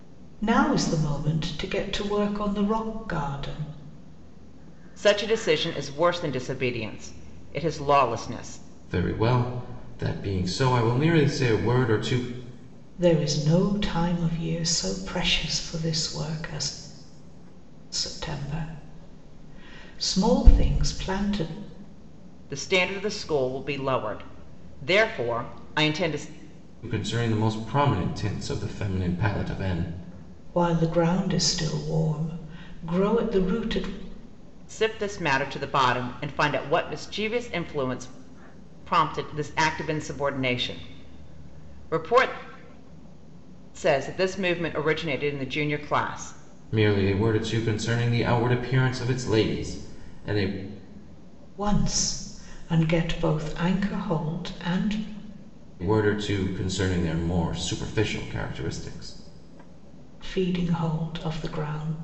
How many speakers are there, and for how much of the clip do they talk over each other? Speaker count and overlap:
3, no overlap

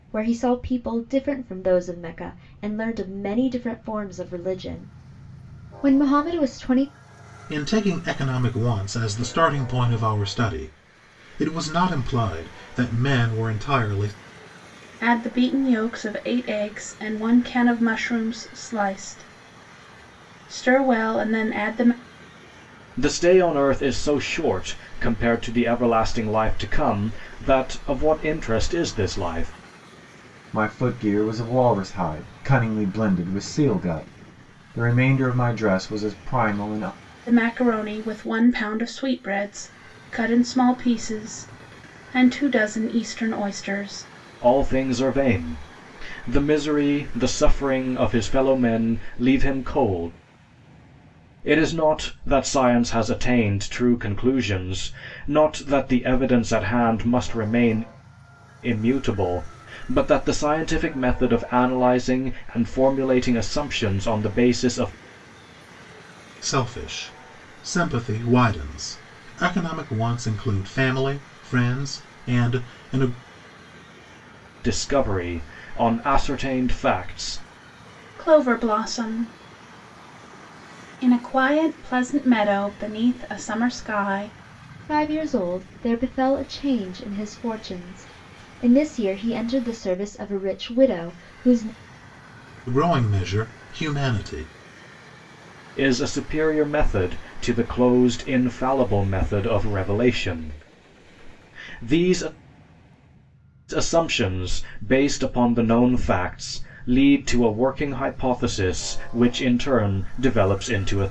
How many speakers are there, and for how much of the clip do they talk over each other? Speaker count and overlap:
5, no overlap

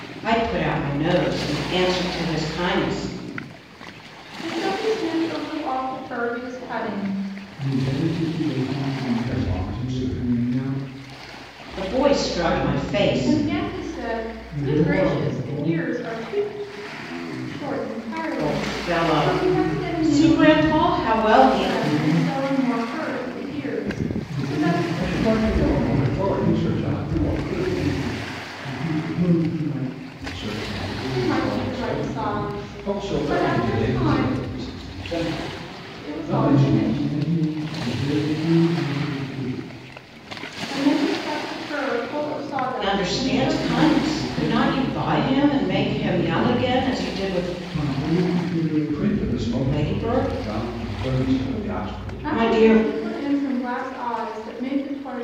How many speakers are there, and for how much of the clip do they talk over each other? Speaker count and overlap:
4, about 48%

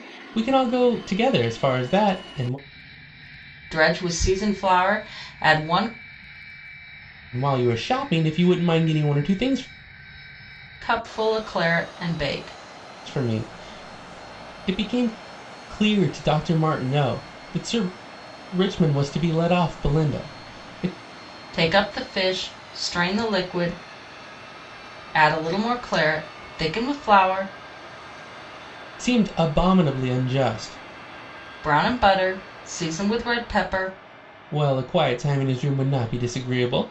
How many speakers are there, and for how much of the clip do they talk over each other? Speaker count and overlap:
2, no overlap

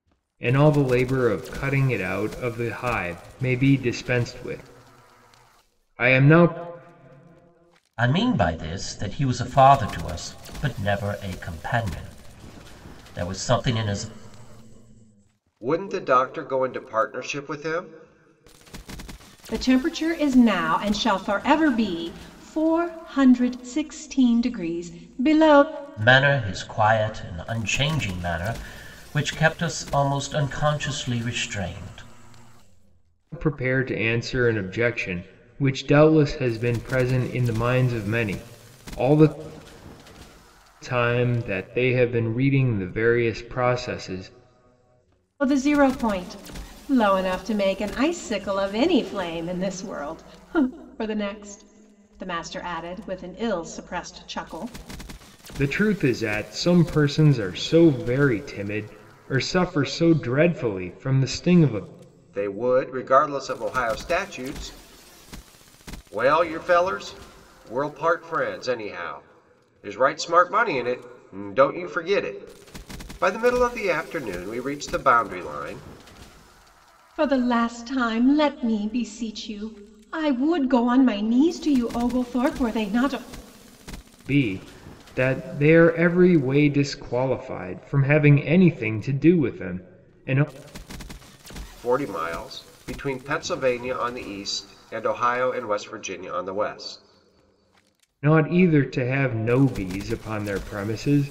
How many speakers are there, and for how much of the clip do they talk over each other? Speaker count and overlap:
4, no overlap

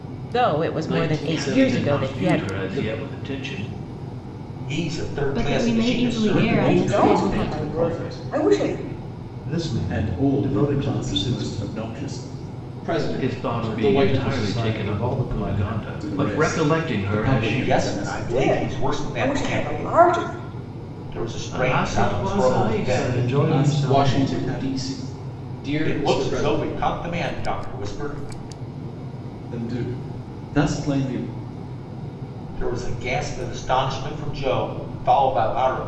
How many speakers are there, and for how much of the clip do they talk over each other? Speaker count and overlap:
8, about 49%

